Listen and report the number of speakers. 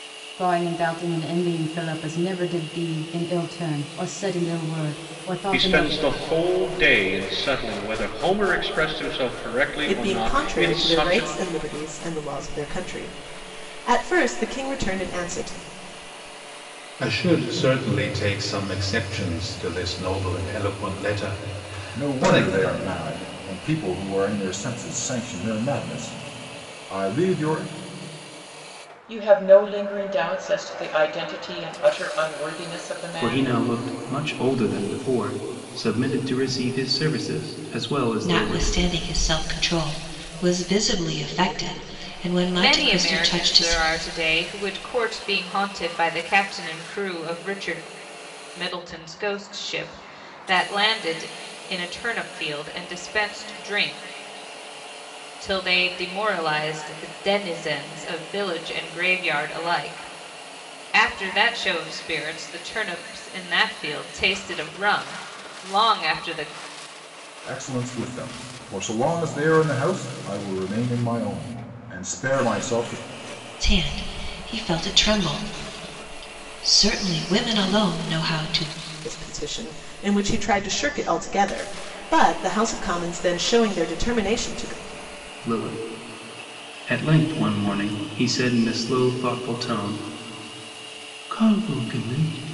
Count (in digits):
9